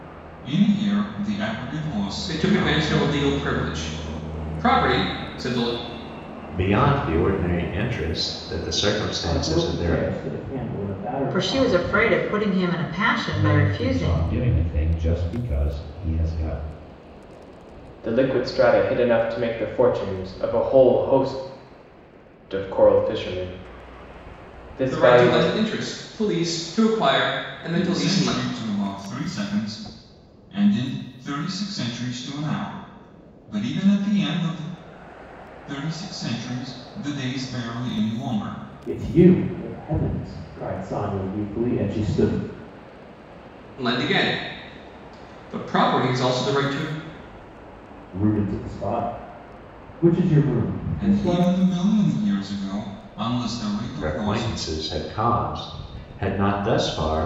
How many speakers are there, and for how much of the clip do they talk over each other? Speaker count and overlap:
7, about 11%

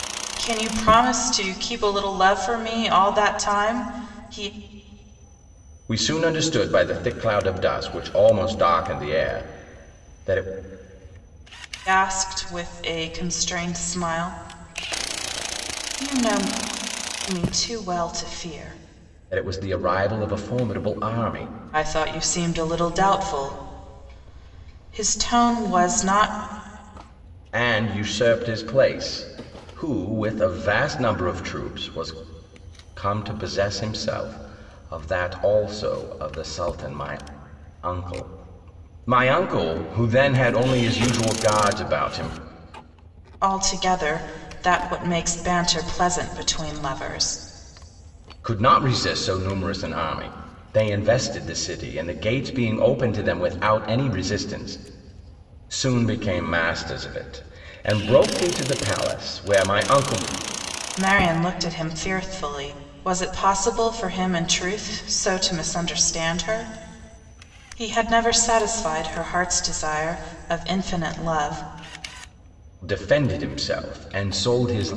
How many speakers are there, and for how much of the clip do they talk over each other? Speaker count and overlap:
2, no overlap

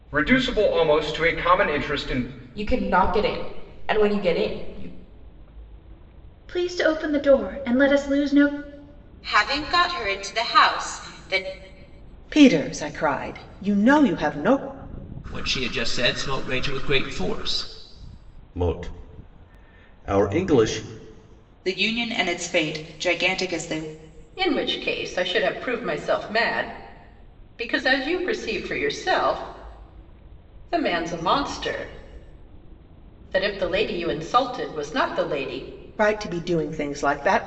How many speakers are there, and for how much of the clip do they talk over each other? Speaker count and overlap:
9, no overlap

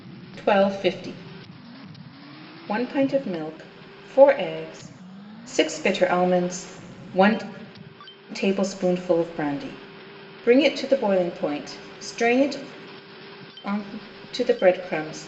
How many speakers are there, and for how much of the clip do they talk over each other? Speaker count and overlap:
1, no overlap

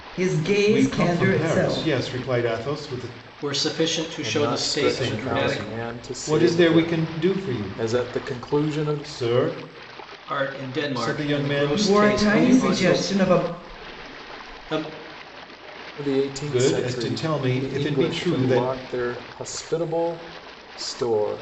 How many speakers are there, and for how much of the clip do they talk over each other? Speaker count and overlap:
4, about 51%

